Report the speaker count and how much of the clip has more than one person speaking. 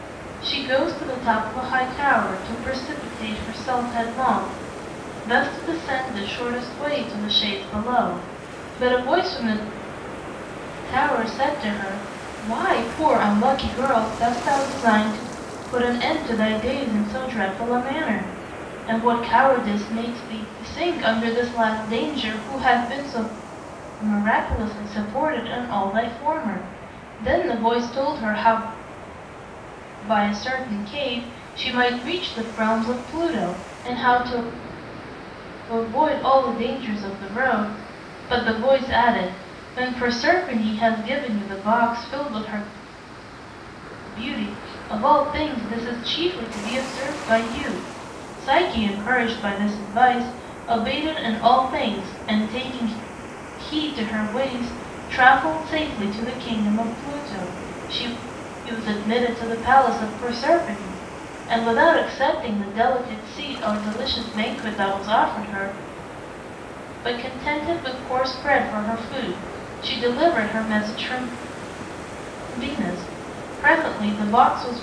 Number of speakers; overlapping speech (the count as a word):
one, no overlap